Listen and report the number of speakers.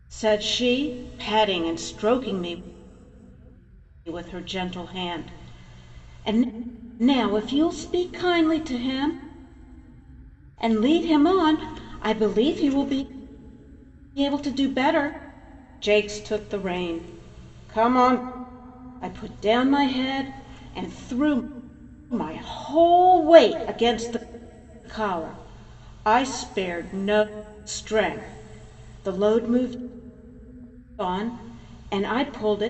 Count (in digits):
1